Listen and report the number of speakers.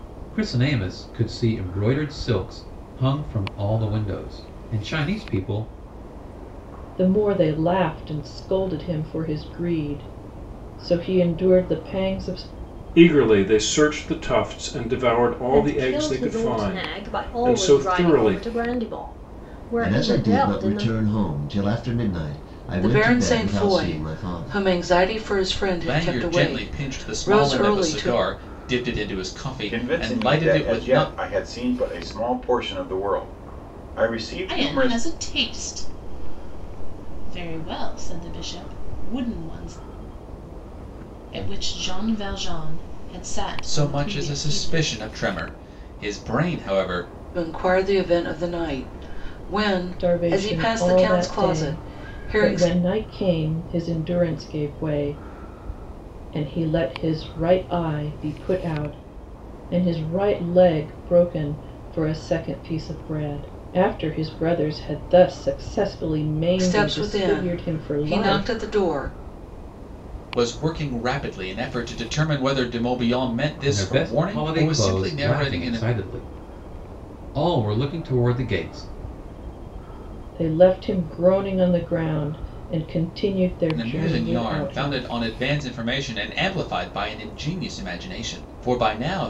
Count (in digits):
9